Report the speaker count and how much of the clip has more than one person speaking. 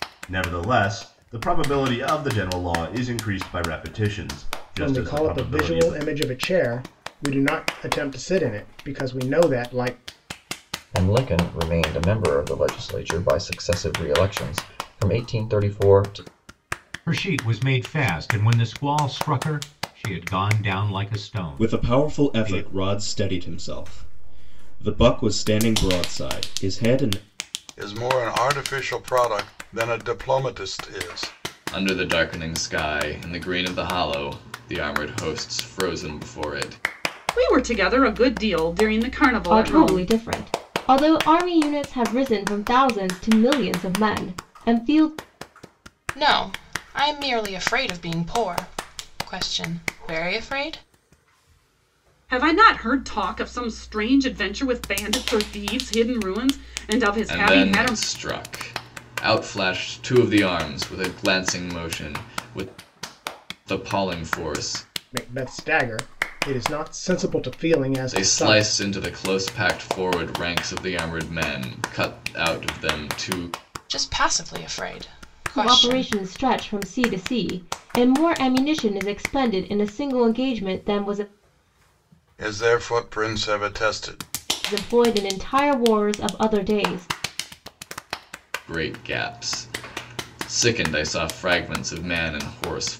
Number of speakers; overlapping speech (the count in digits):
10, about 5%